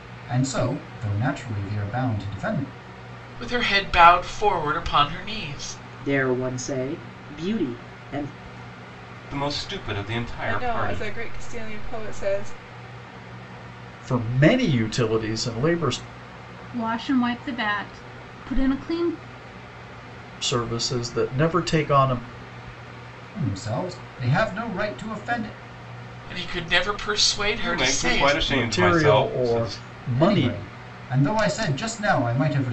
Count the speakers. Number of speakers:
7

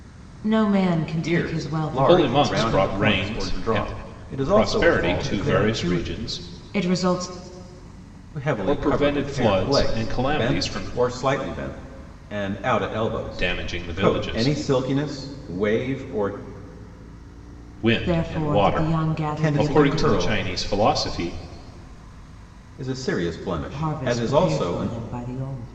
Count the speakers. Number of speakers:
3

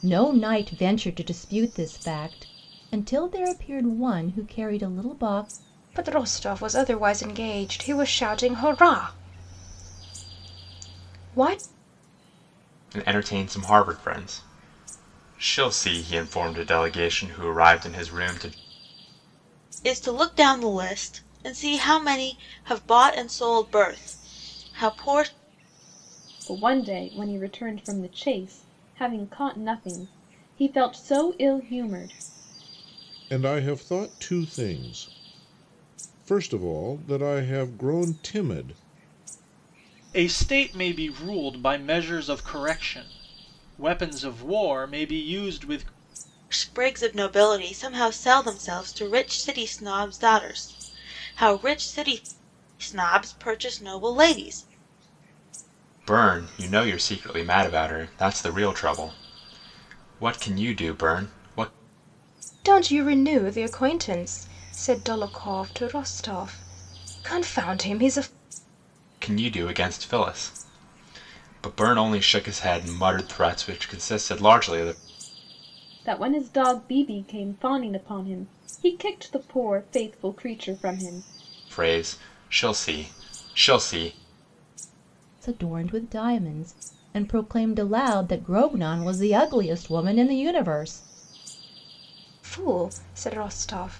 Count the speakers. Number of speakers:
7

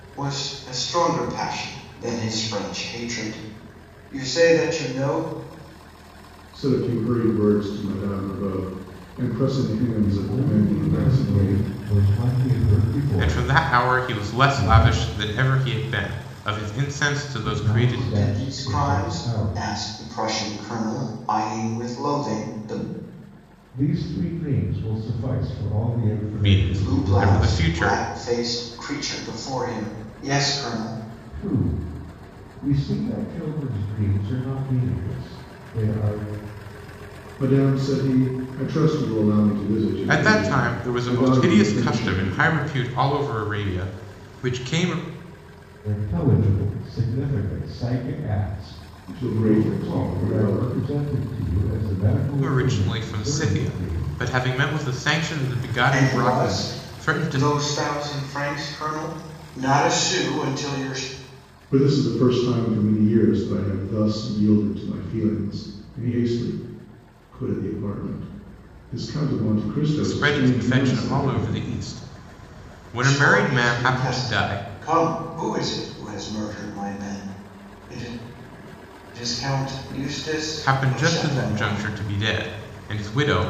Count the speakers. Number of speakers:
4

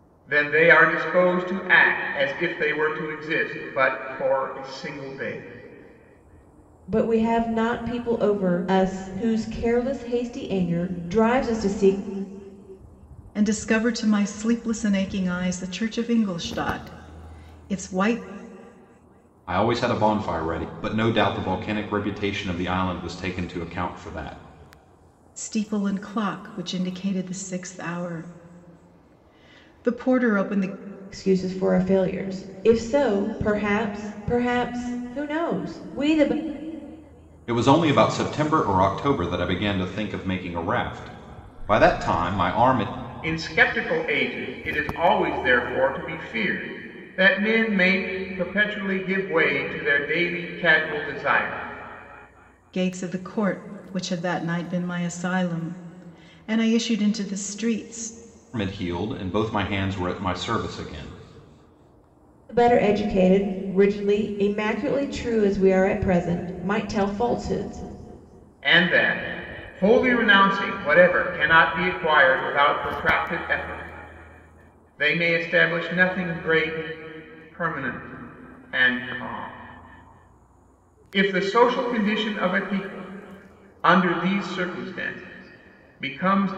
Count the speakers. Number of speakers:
4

